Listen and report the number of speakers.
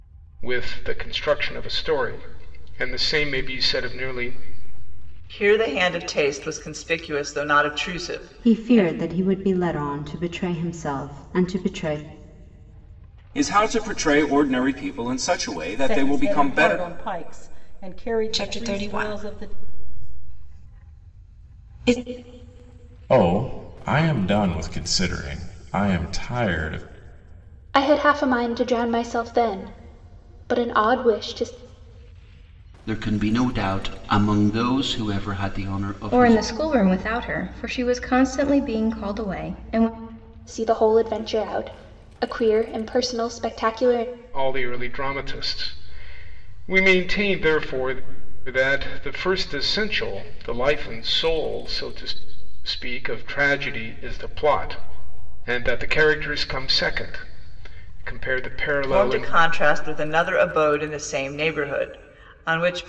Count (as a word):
ten